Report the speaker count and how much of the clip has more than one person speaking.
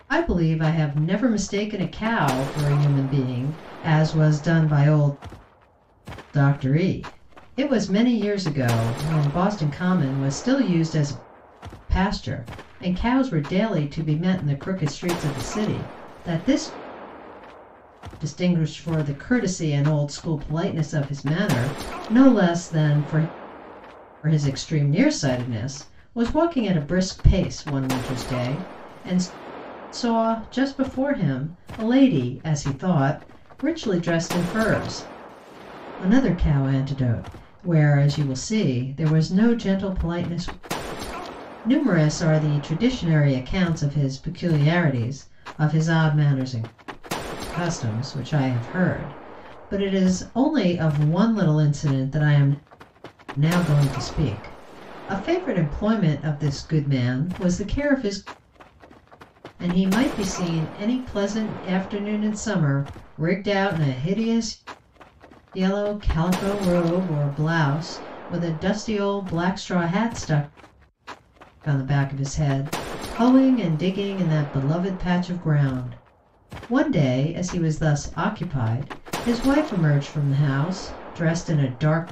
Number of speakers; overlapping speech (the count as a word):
one, no overlap